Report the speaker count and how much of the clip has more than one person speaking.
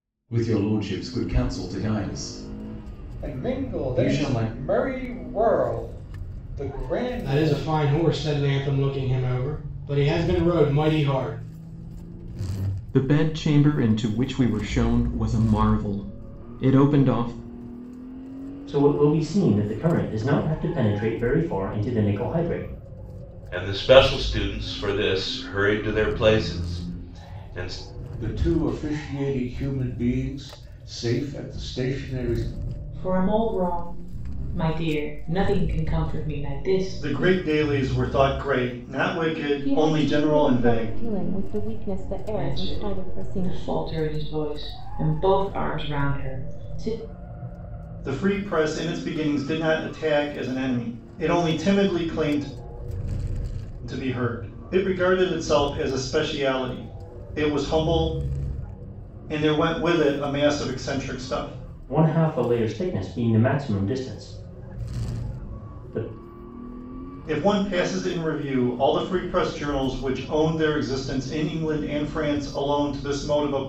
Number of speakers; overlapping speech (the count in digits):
10, about 7%